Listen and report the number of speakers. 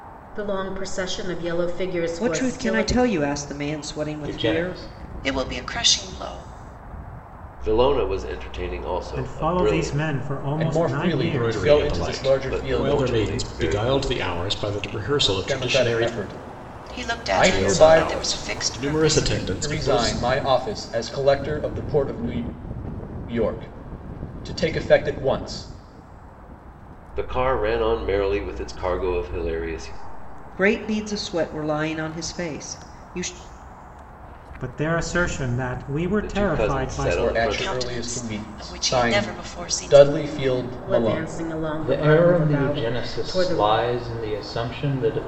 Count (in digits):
8